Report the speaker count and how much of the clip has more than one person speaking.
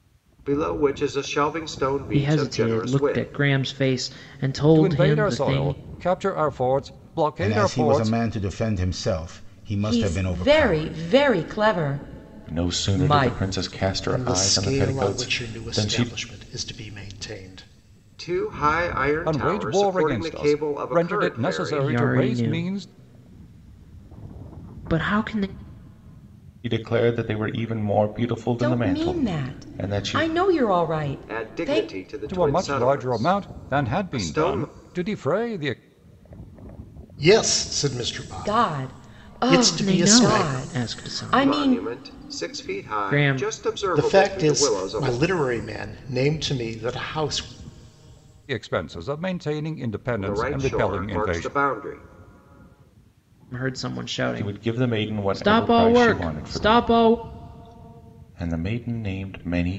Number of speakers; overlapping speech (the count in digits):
7, about 45%